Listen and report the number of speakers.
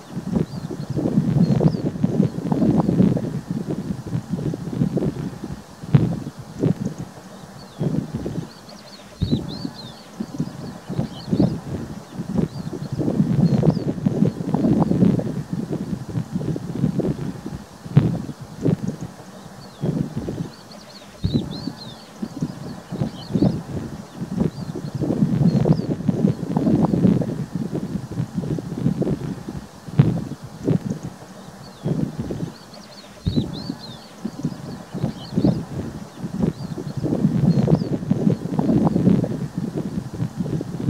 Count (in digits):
0